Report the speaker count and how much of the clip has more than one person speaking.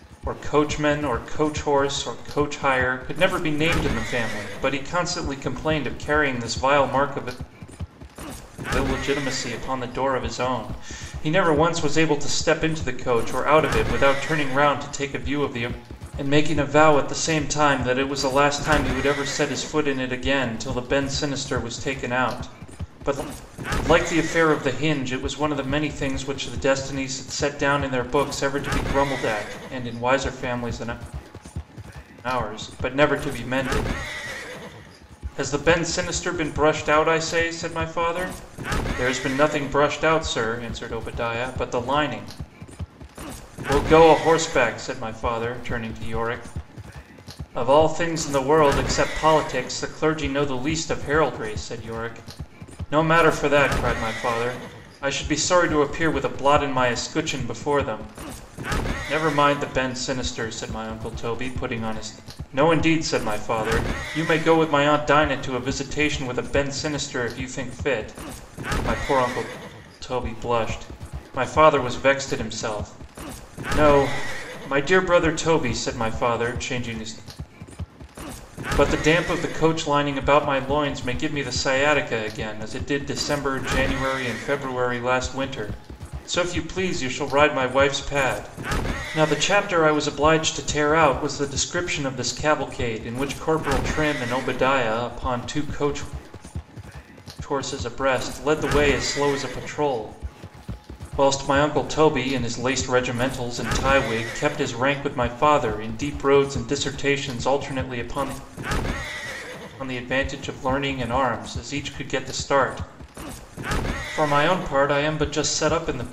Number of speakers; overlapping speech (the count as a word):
one, no overlap